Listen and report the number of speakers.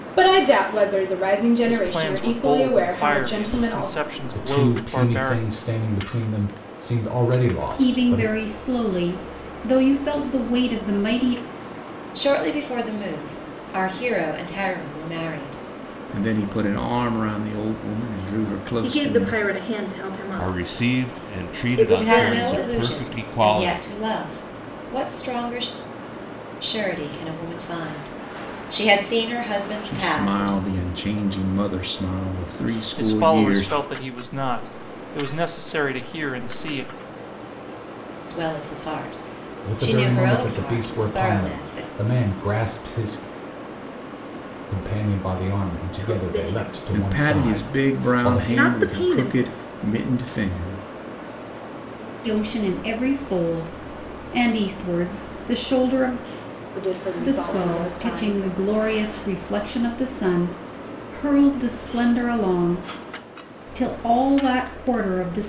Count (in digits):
8